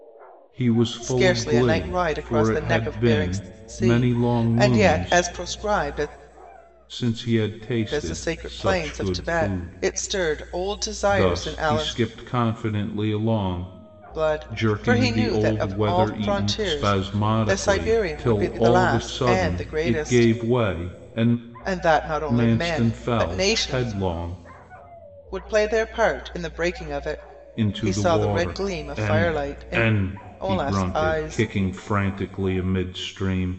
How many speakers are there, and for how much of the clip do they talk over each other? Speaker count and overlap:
2, about 54%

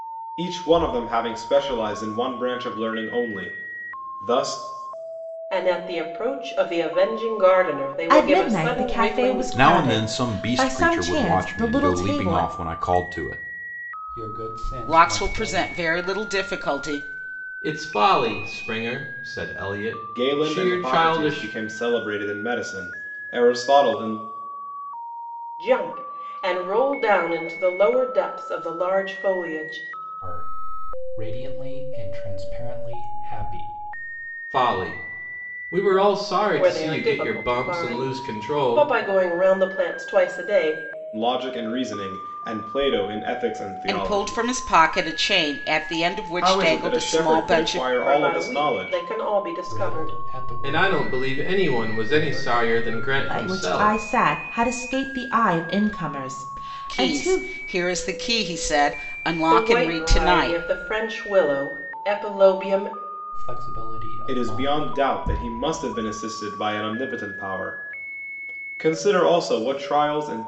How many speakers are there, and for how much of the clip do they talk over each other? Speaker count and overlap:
7, about 27%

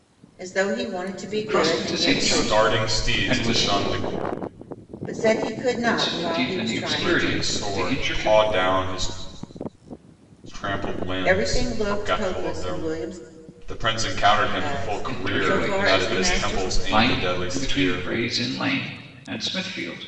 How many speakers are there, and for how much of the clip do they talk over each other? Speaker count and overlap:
3, about 48%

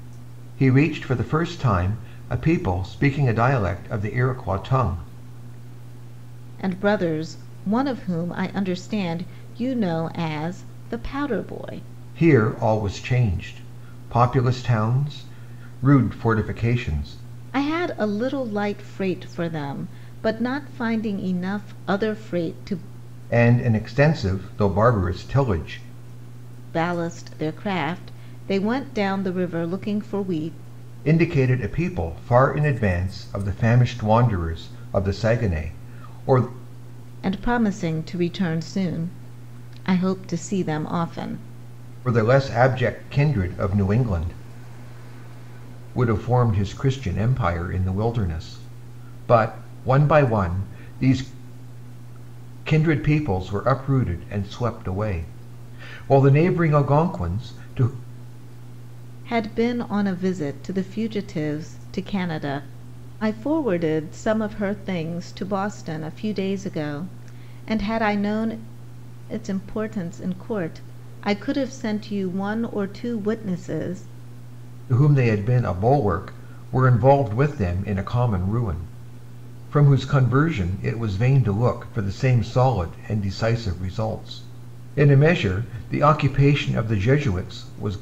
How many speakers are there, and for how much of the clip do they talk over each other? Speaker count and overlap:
2, no overlap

